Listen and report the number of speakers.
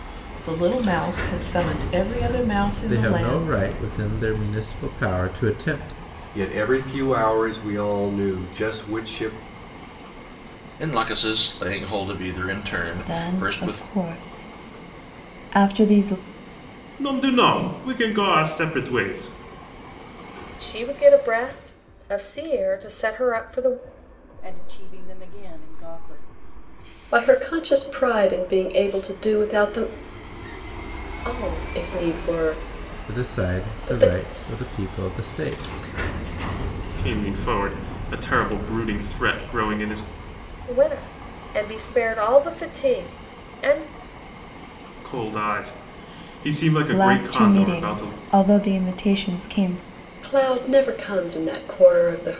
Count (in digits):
9